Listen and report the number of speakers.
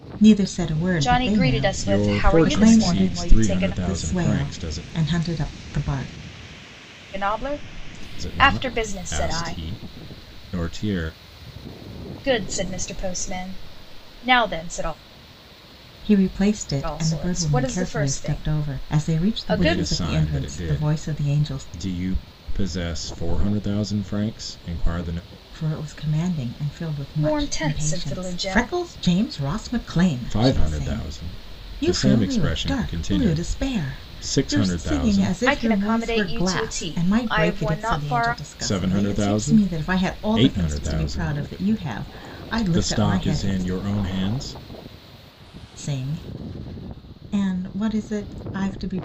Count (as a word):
three